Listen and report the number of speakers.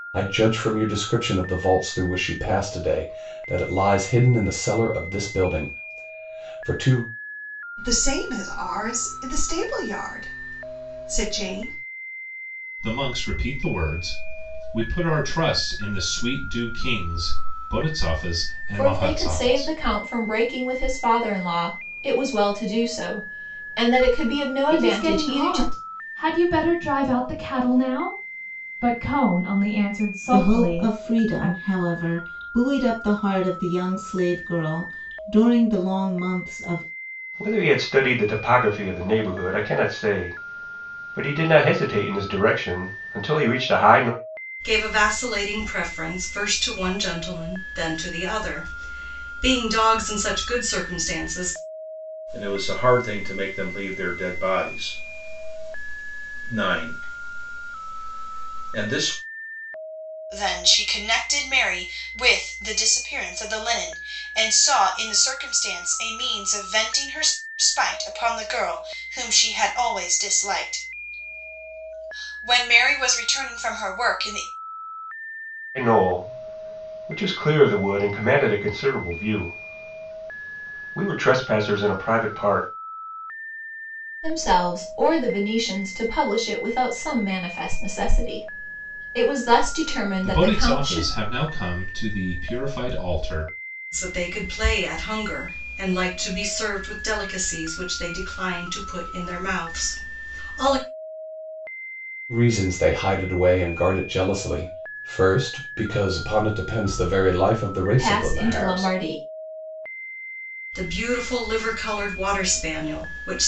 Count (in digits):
10